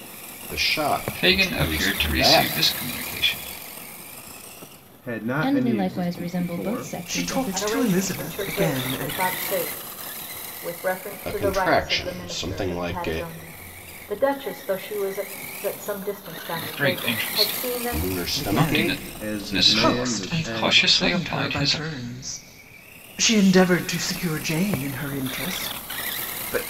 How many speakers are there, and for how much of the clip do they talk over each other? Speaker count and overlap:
six, about 47%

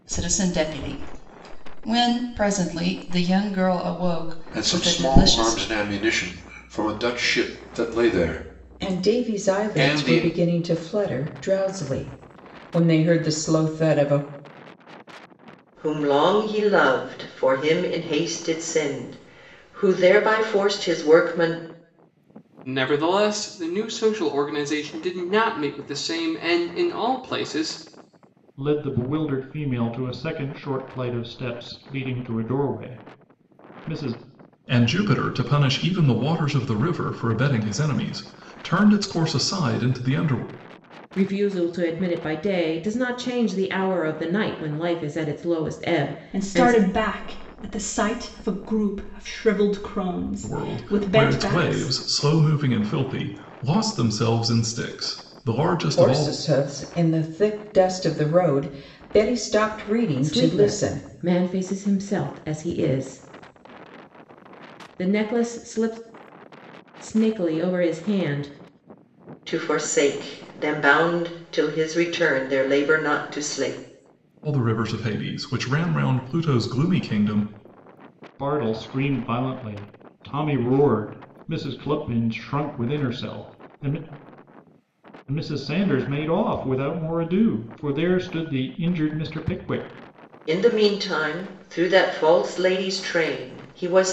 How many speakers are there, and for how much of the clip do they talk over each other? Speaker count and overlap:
nine, about 6%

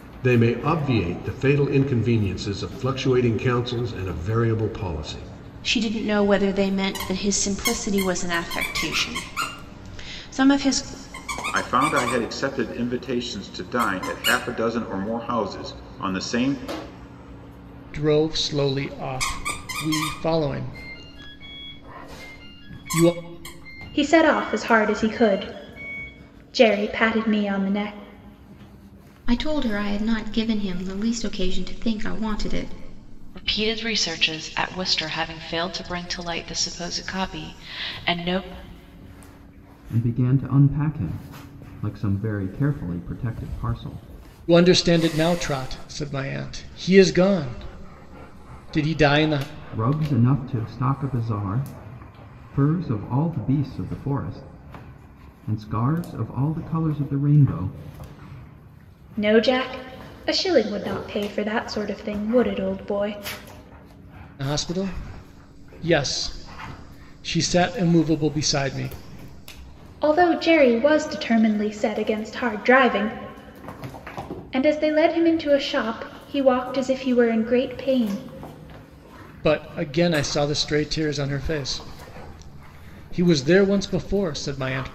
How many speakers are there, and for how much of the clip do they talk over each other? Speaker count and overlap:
eight, no overlap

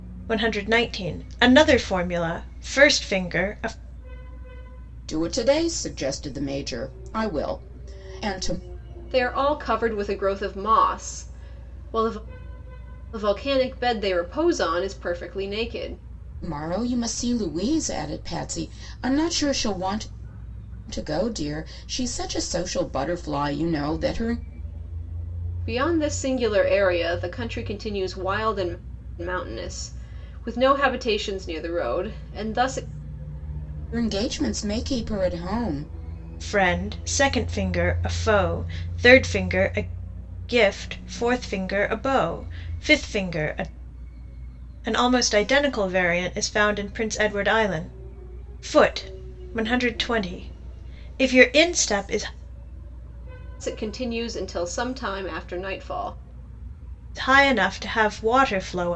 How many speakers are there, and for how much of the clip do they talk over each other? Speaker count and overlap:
three, no overlap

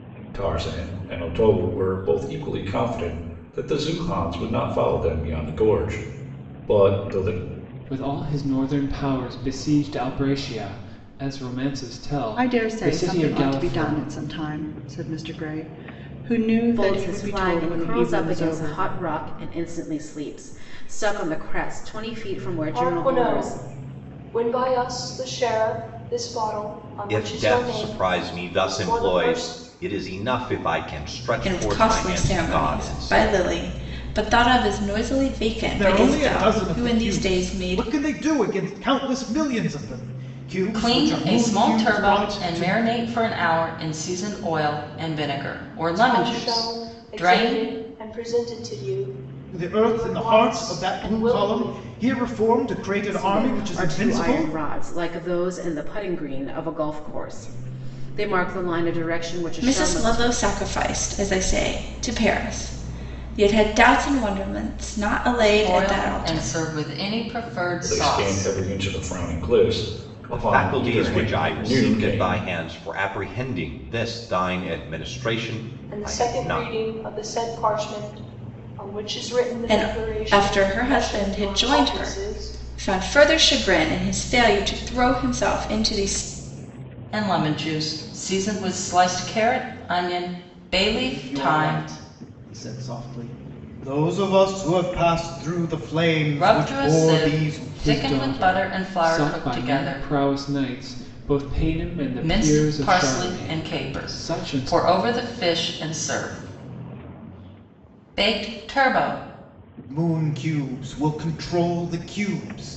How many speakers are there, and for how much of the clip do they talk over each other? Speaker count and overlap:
nine, about 31%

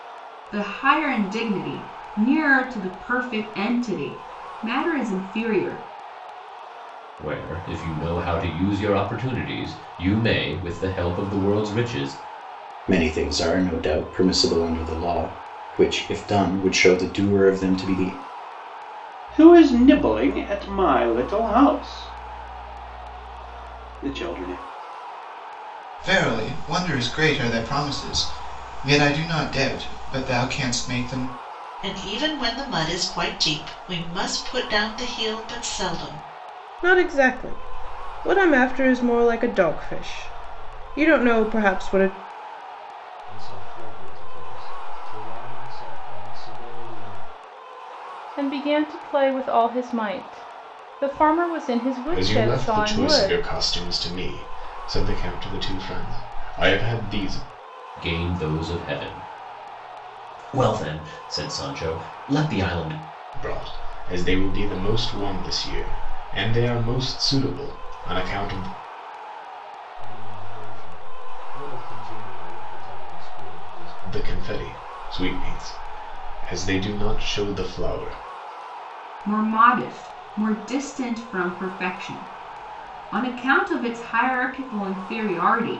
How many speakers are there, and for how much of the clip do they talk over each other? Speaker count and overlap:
ten, about 2%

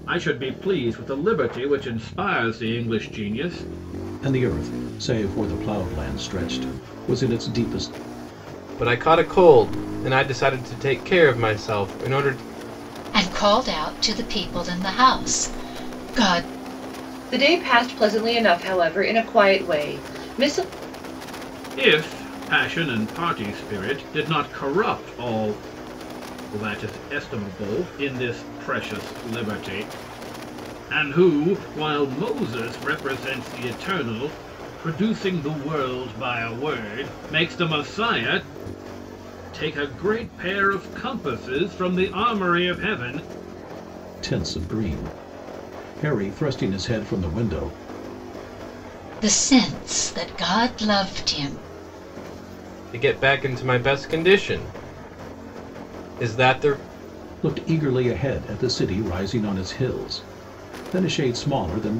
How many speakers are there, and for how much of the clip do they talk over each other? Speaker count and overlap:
five, no overlap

